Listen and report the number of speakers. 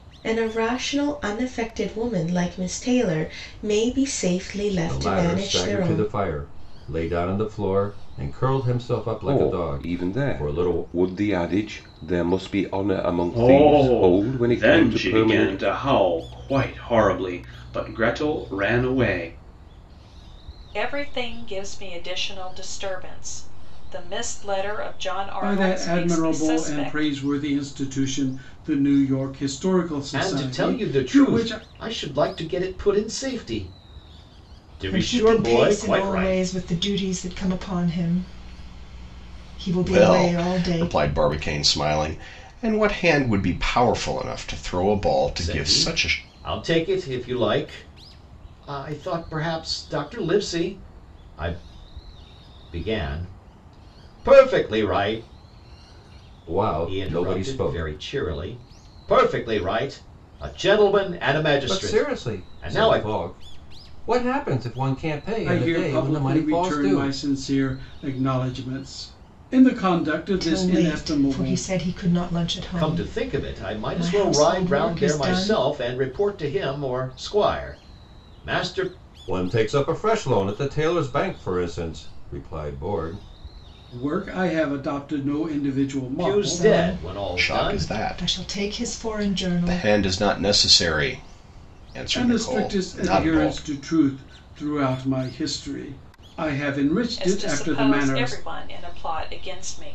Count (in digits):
9